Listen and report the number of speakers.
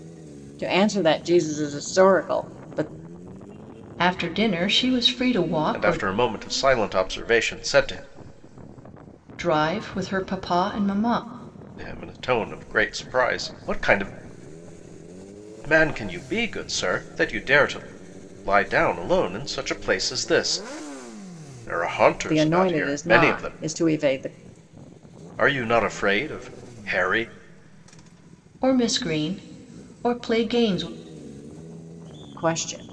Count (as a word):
three